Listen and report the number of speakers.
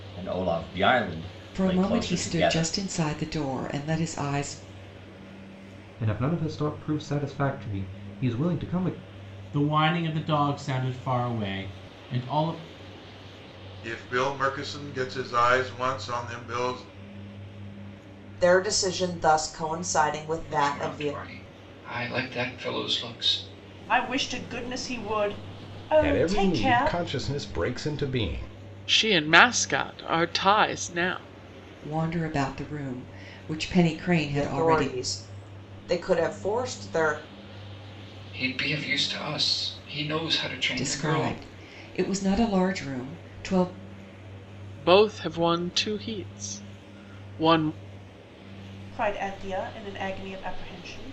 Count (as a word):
ten